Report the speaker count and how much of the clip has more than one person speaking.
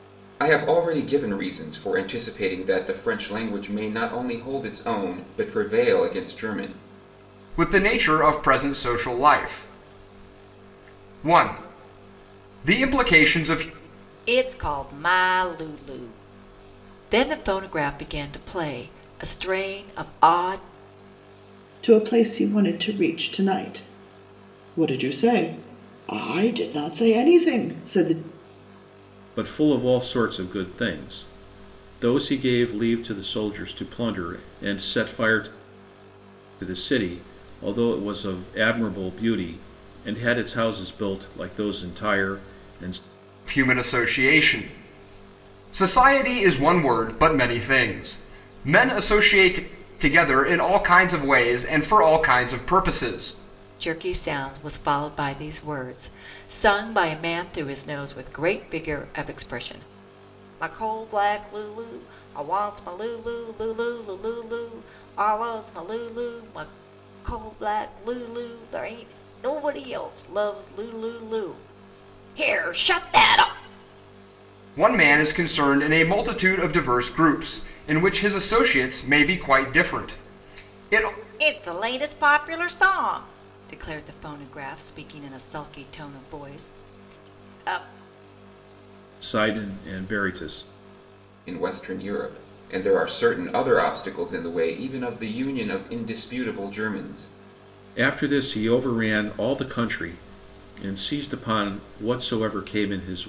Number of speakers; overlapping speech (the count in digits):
5, no overlap